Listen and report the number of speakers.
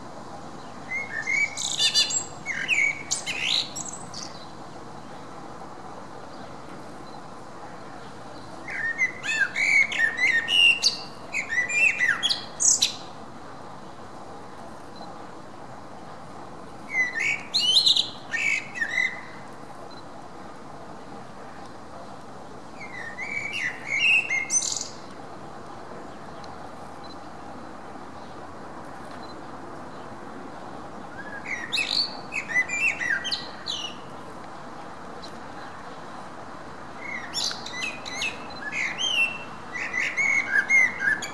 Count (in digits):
0